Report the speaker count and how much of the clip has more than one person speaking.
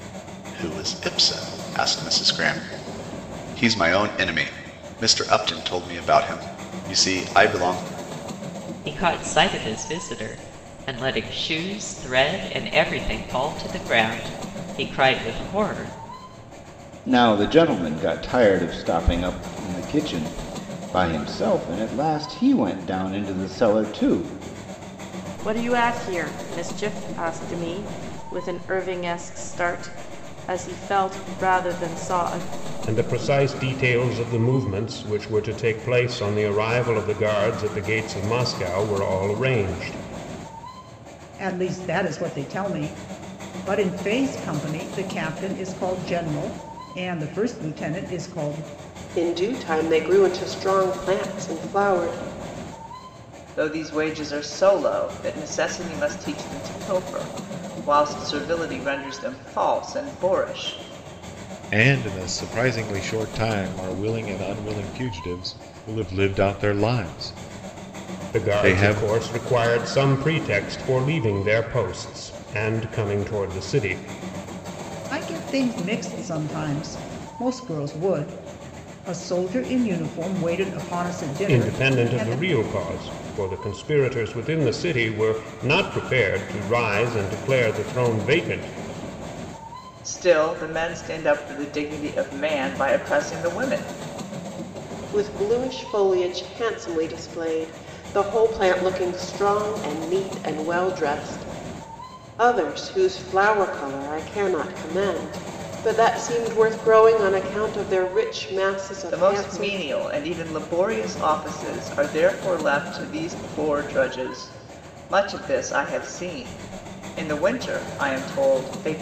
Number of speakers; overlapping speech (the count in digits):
9, about 2%